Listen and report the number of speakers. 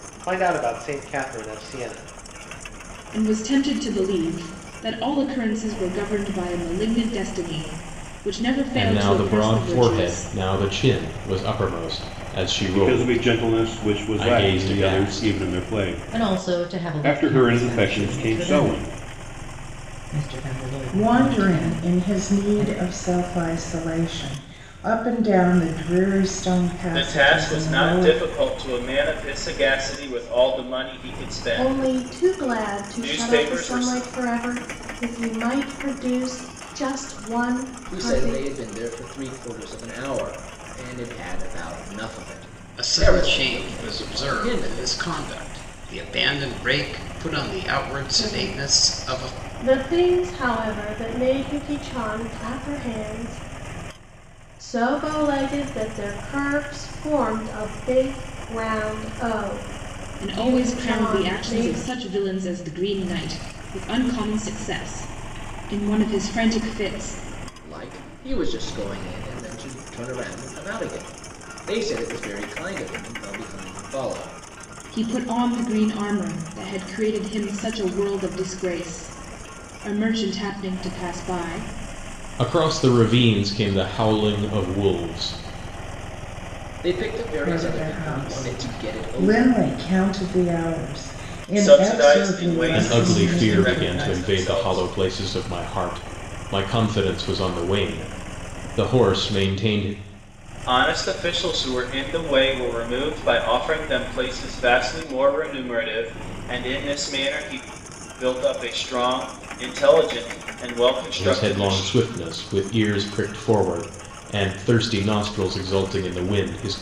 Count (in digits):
10